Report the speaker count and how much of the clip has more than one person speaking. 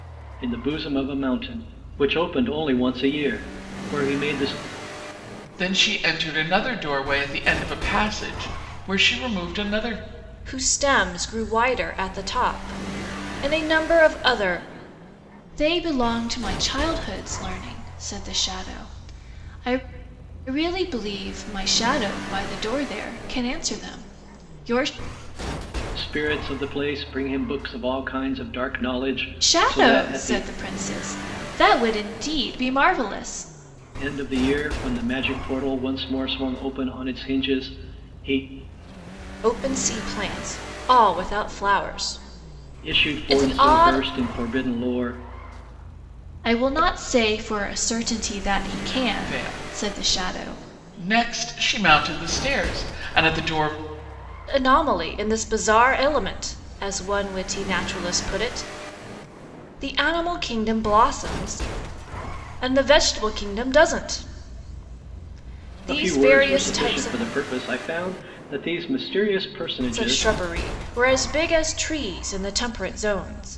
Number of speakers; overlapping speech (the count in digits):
4, about 7%